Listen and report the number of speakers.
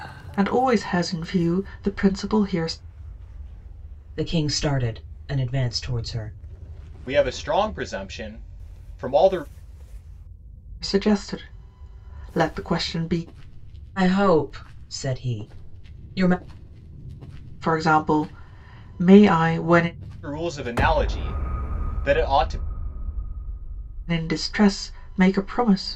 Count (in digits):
3